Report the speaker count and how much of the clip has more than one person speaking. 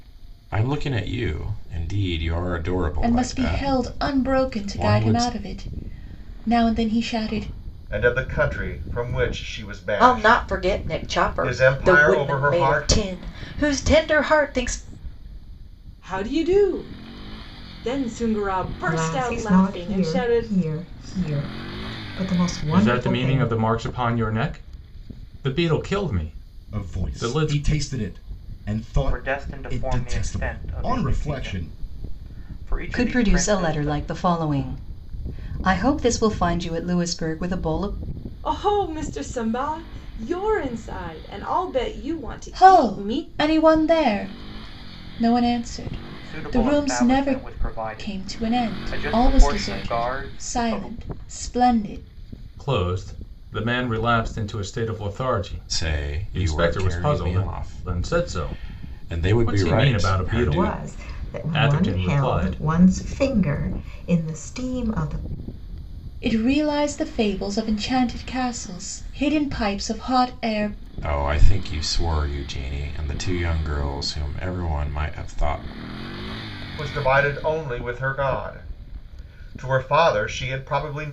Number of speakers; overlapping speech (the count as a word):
ten, about 30%